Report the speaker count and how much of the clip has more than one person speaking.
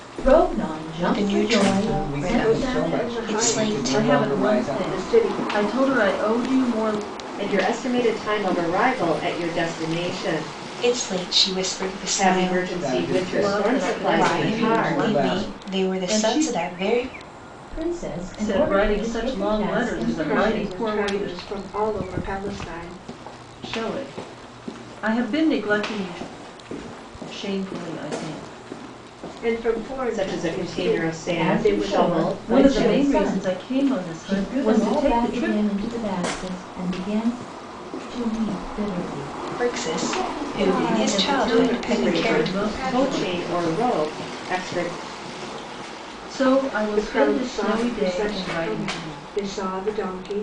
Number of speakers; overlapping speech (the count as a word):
six, about 46%